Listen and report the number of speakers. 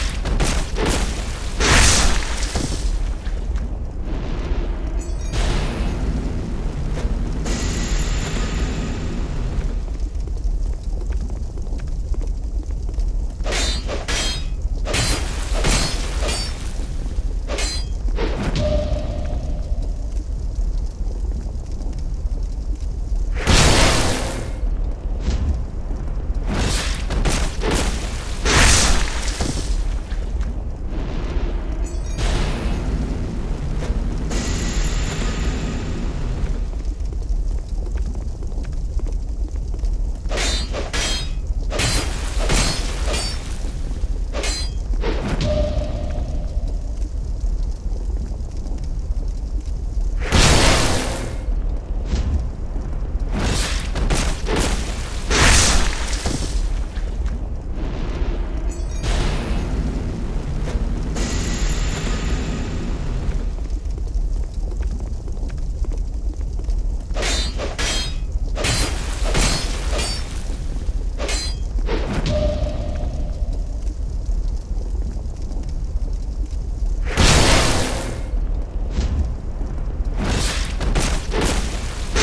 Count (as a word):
zero